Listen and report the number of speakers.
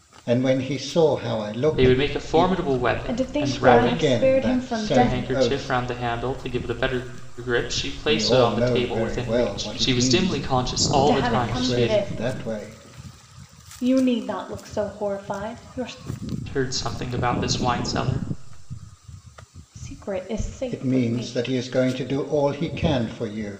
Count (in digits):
3